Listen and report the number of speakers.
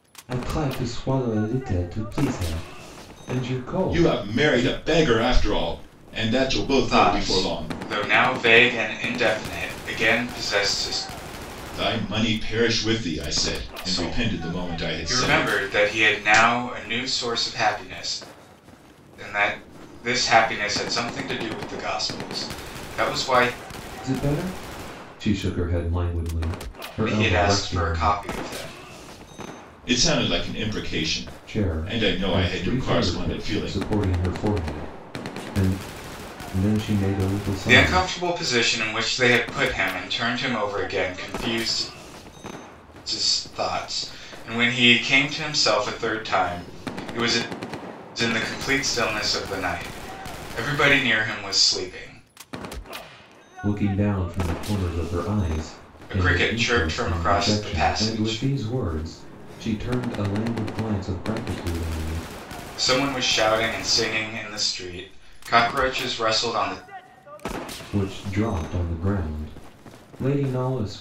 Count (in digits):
3